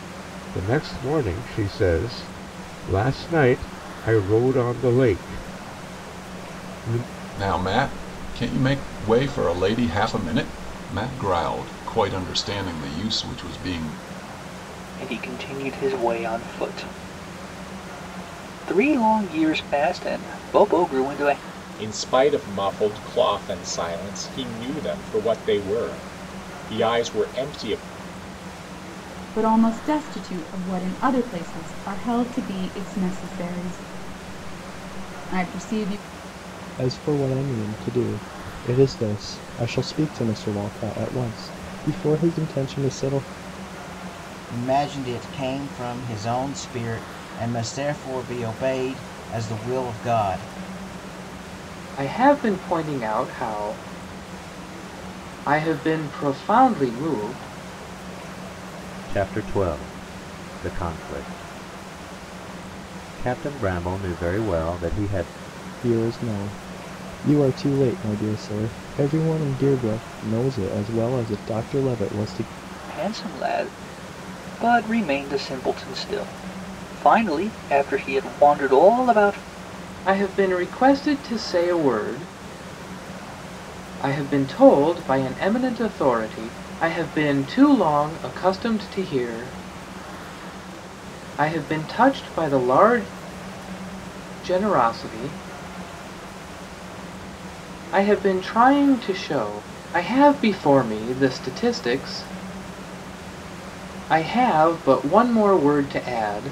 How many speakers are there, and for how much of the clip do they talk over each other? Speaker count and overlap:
nine, no overlap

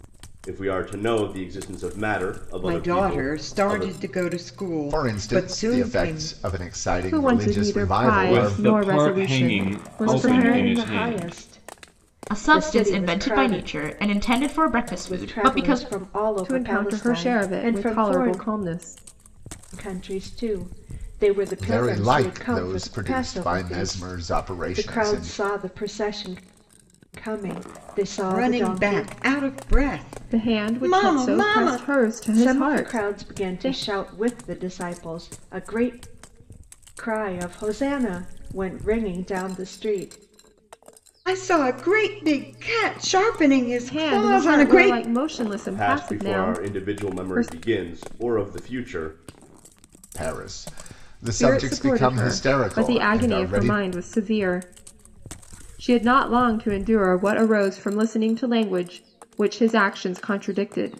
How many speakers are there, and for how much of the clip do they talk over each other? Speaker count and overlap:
seven, about 41%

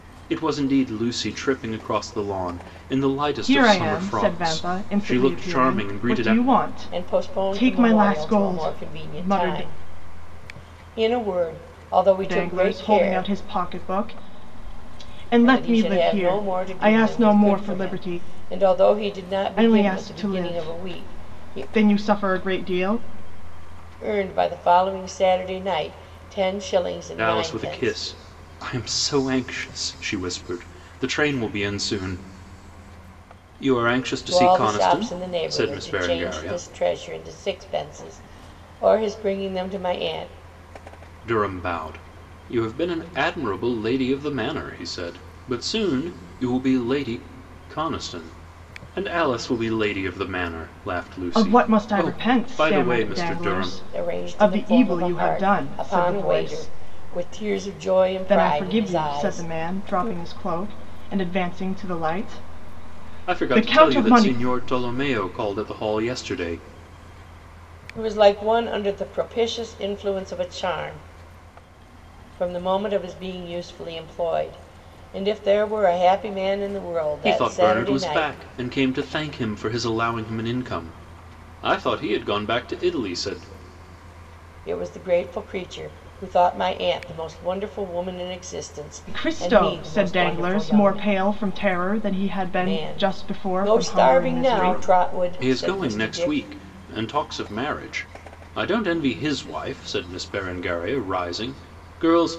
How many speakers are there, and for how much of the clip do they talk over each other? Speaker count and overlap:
three, about 30%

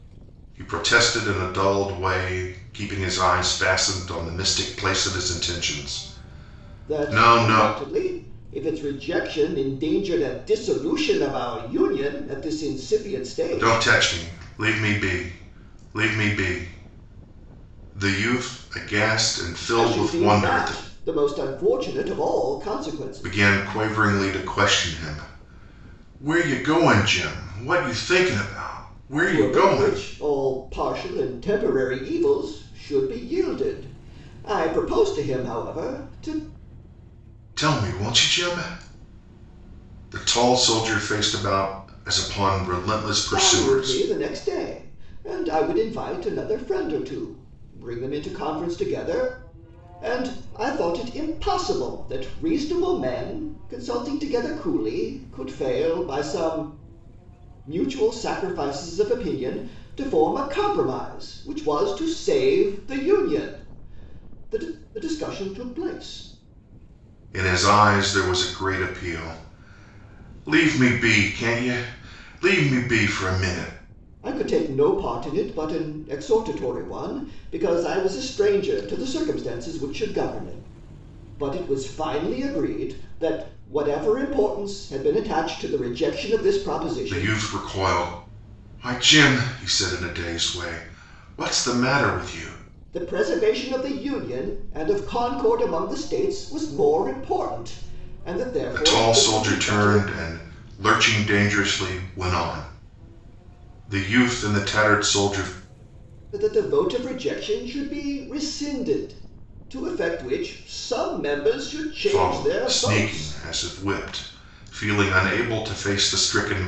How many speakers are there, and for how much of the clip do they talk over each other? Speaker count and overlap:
two, about 6%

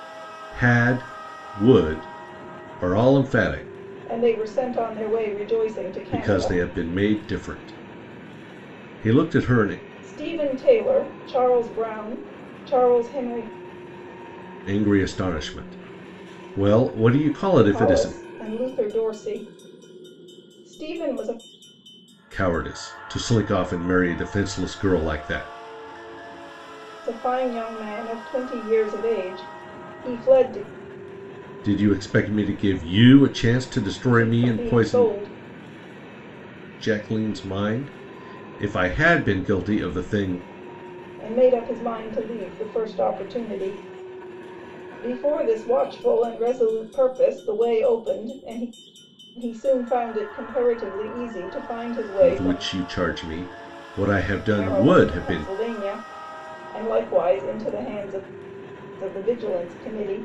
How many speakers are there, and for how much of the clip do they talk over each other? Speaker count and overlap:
two, about 6%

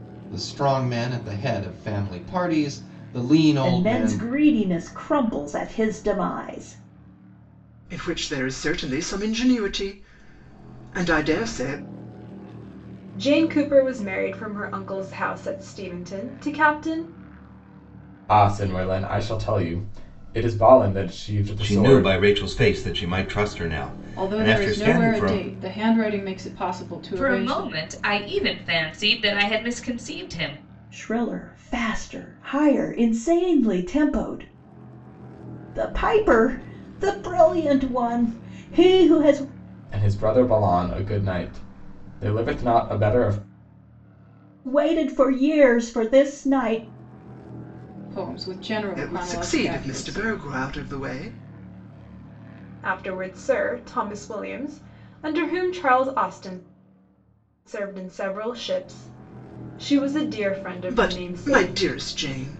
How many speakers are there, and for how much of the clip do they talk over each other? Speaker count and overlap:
eight, about 9%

